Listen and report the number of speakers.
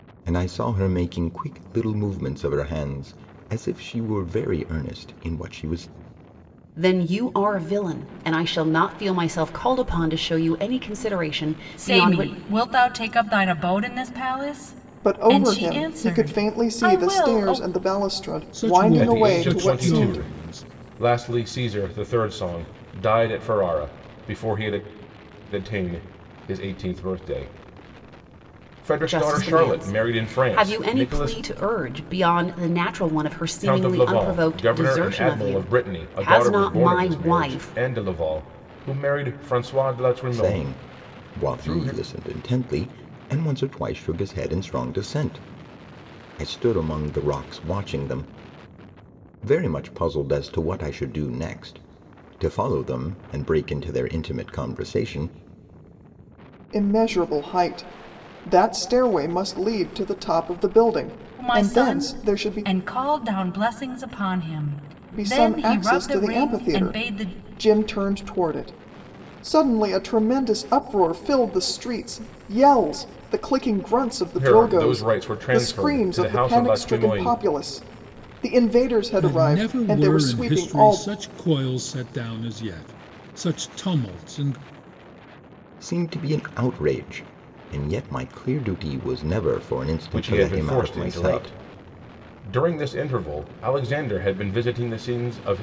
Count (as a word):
six